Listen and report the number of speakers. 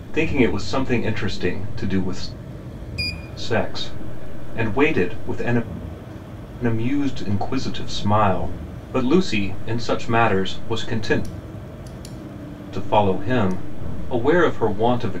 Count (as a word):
one